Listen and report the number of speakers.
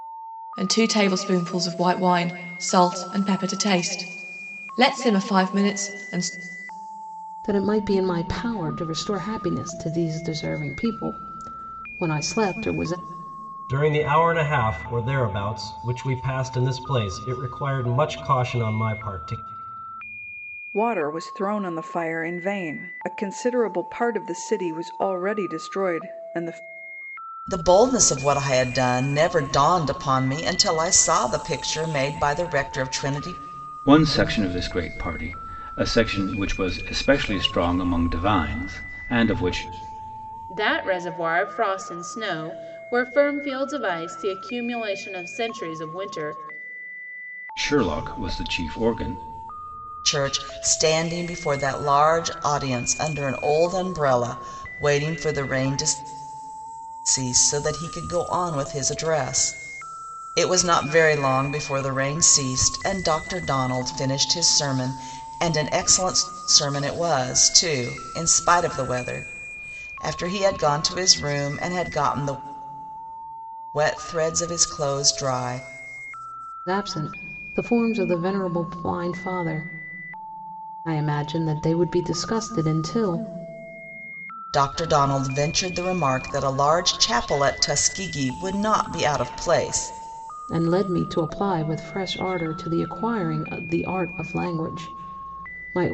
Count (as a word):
seven